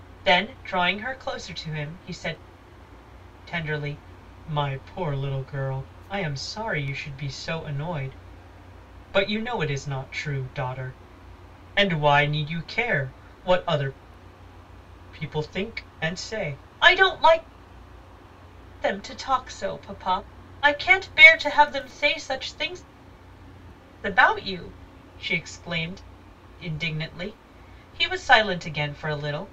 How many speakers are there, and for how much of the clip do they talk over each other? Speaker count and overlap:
one, no overlap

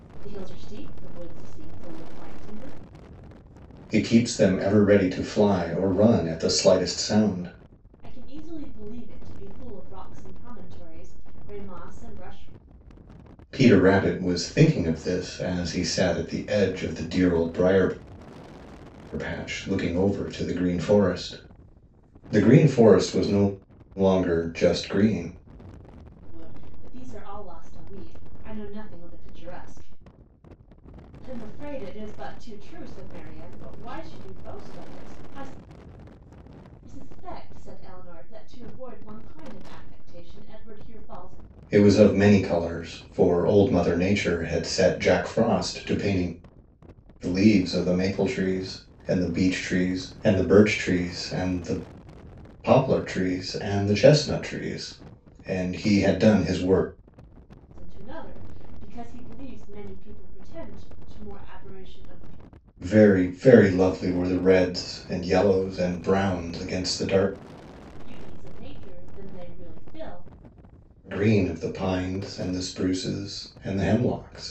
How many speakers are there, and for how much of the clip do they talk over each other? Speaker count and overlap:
two, no overlap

